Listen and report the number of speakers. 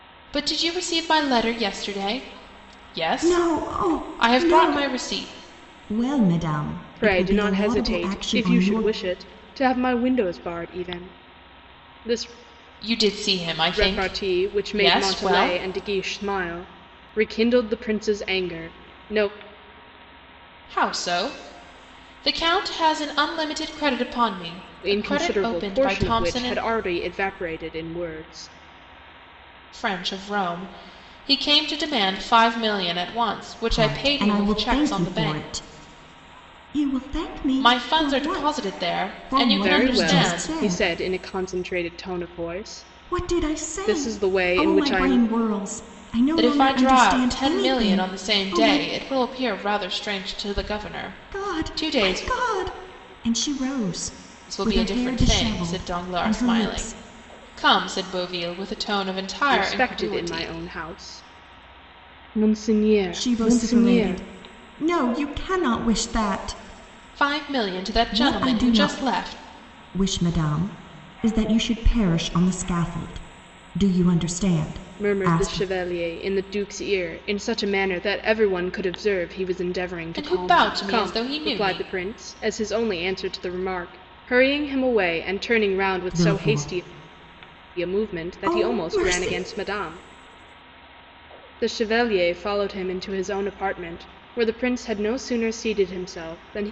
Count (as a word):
three